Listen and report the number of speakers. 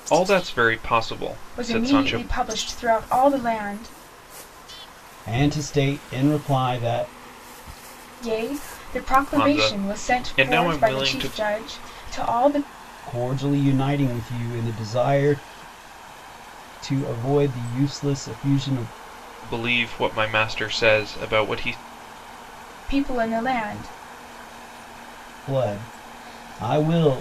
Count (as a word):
three